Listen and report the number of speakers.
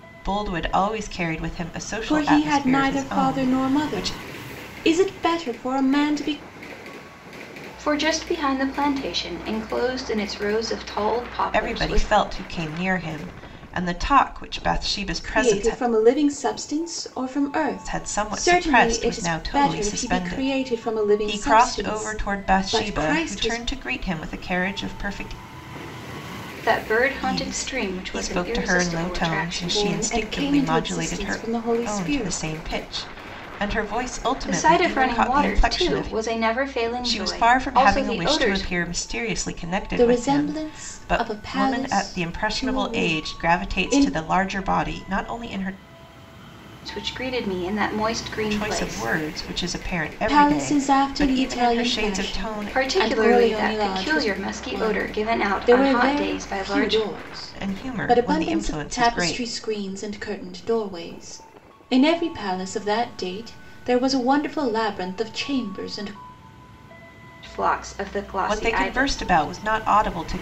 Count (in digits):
3